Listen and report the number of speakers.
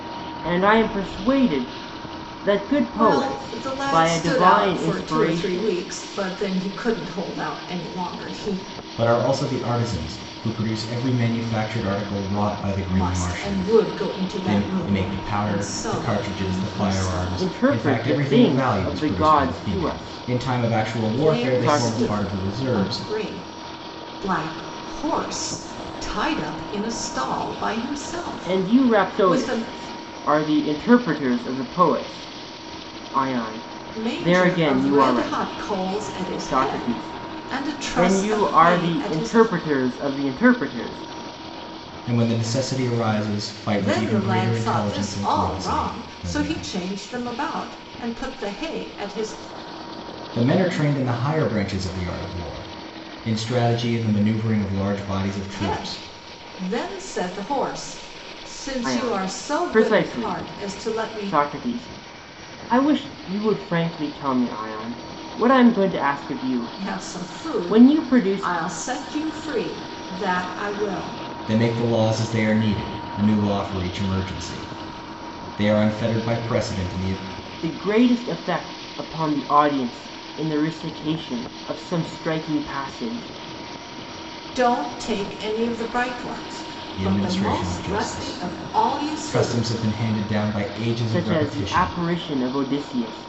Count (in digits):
3